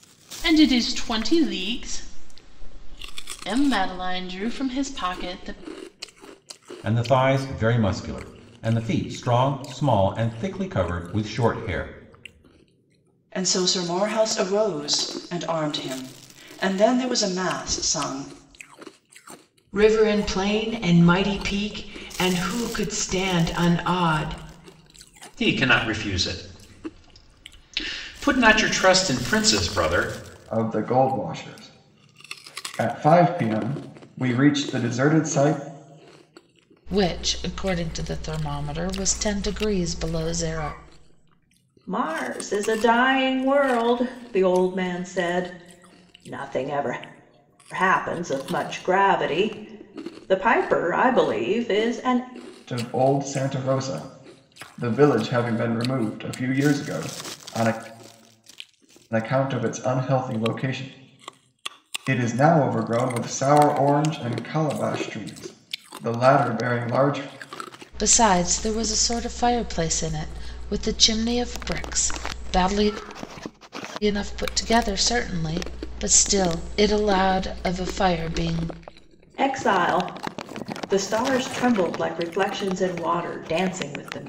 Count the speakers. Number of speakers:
eight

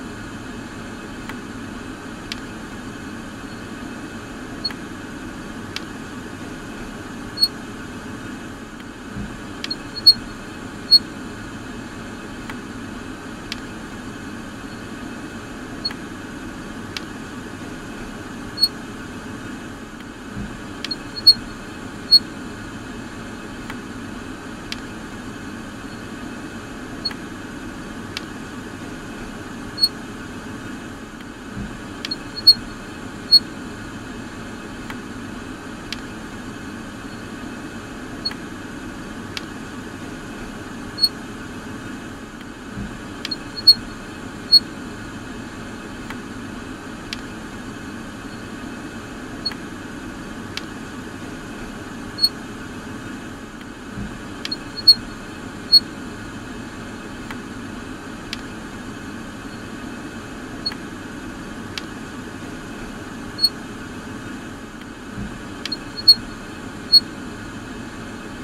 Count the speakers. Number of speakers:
zero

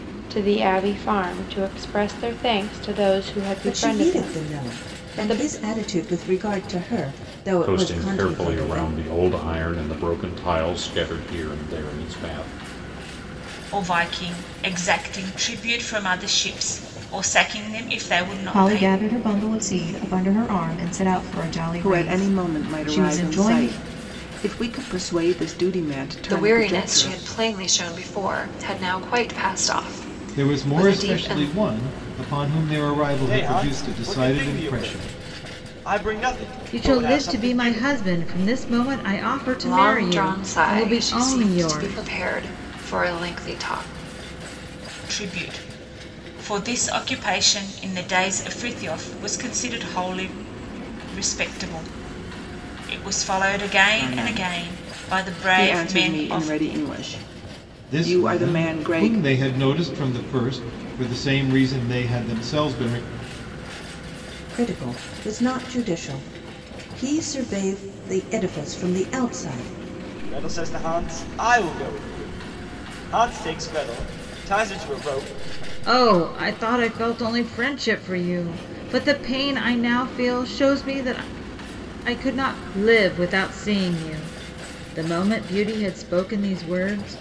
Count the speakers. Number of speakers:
ten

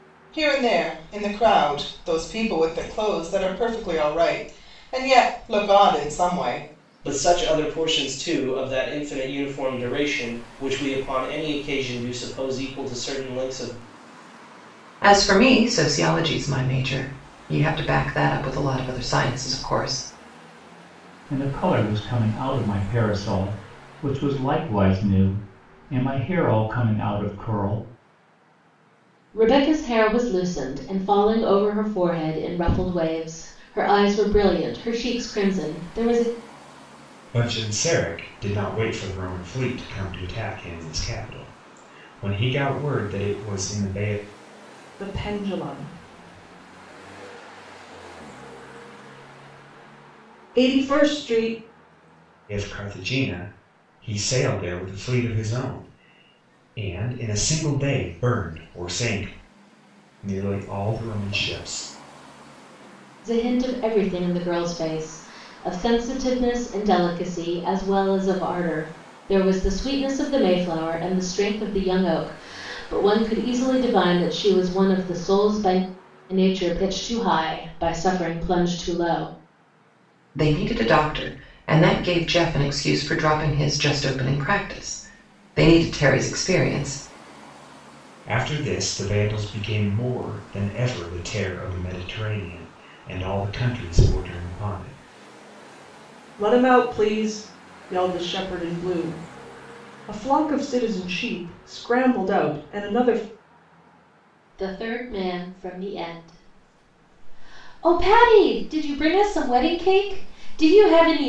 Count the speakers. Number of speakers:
seven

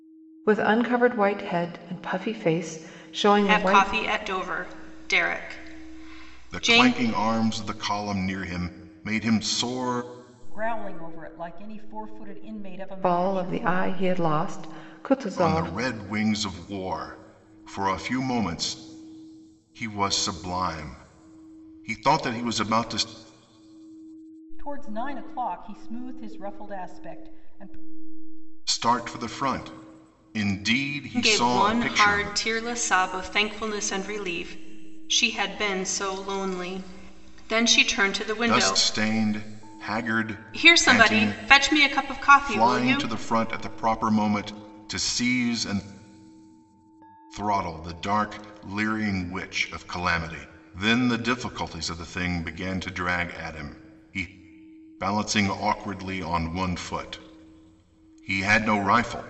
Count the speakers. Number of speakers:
four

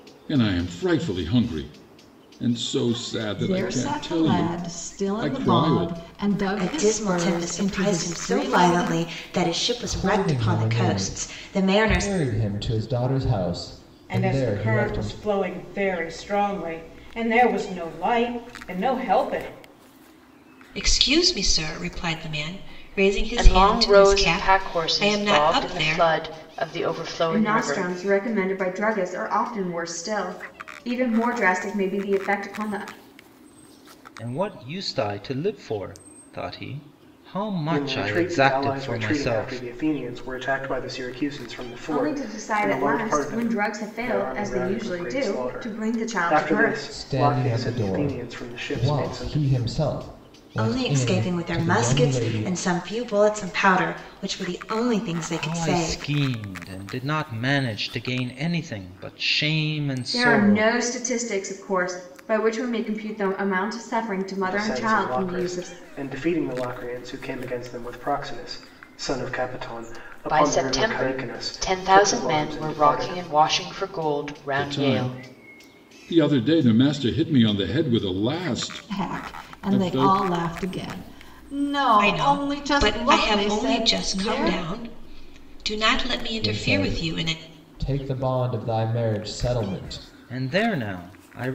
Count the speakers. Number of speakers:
ten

